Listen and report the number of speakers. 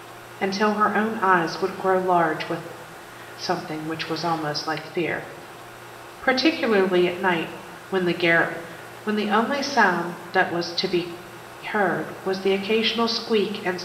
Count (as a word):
one